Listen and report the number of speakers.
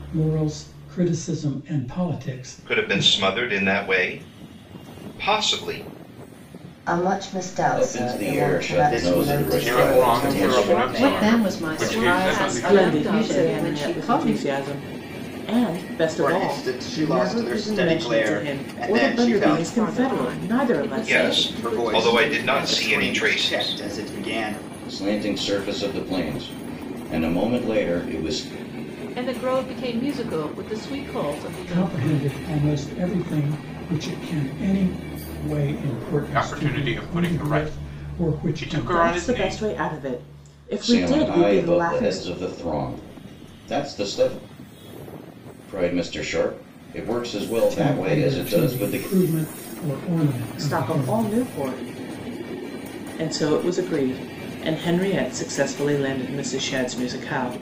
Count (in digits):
9